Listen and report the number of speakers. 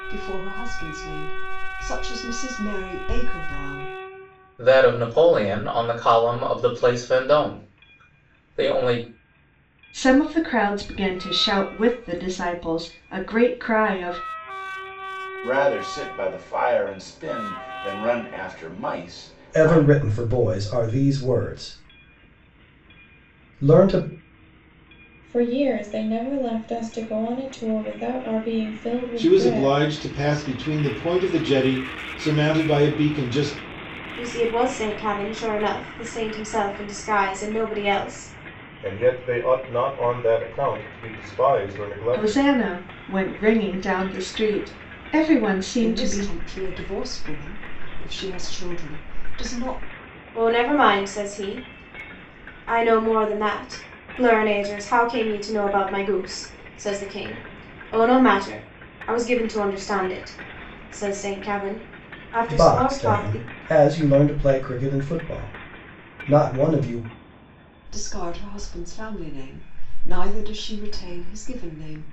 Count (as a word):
nine